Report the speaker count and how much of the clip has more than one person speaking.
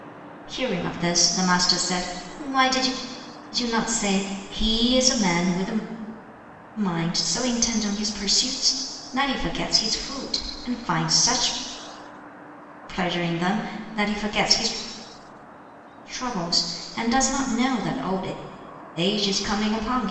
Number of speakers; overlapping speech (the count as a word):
one, no overlap